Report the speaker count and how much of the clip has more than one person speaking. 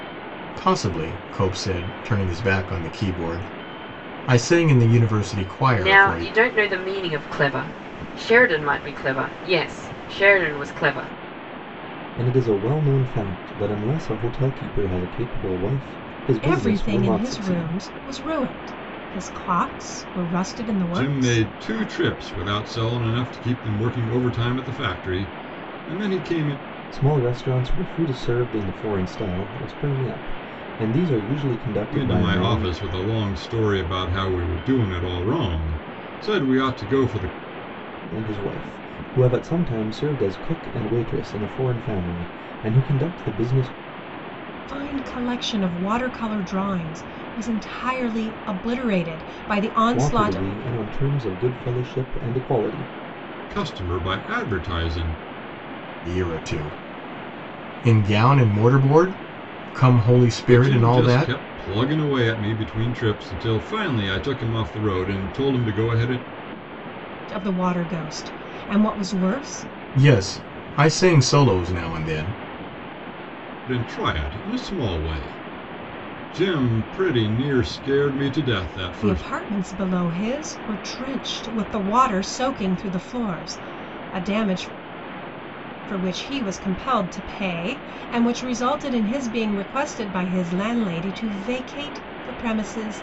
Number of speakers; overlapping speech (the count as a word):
five, about 6%